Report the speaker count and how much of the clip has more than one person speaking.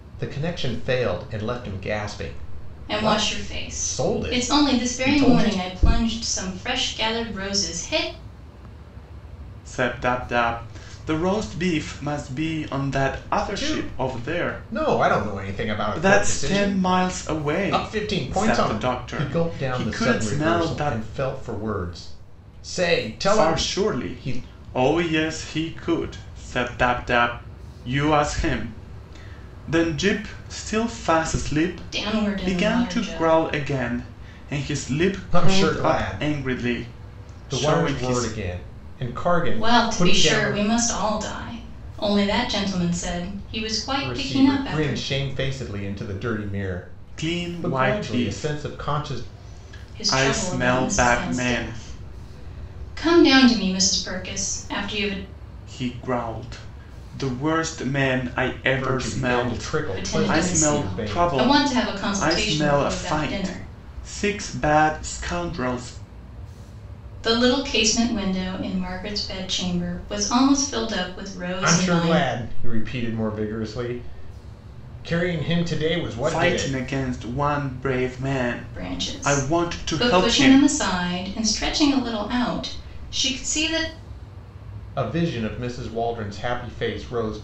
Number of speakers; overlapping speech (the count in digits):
3, about 33%